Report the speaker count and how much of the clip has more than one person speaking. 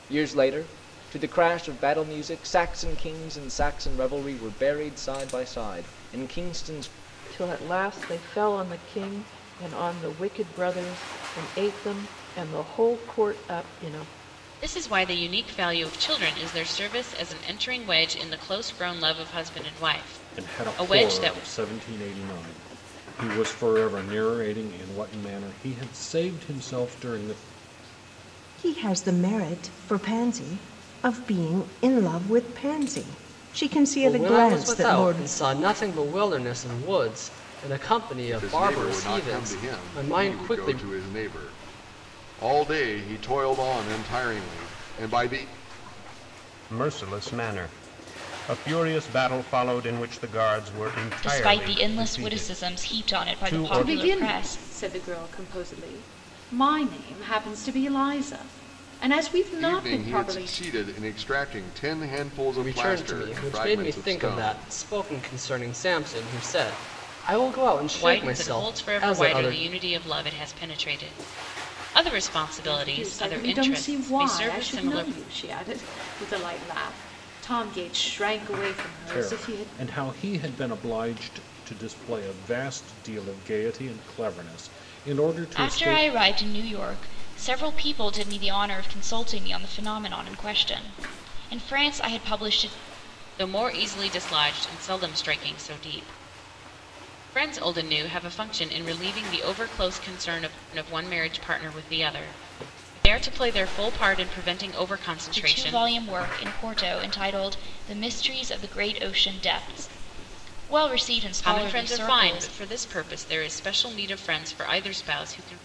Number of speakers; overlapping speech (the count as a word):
ten, about 16%